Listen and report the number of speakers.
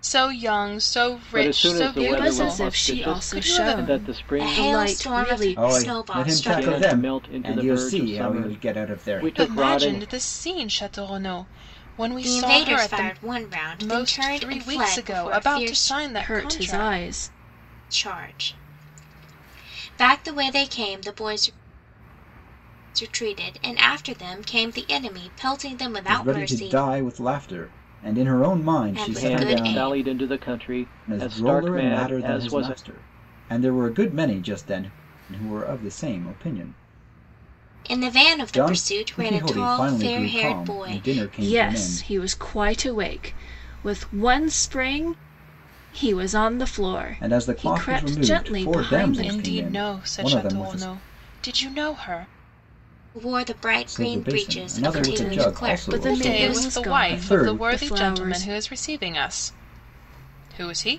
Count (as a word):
five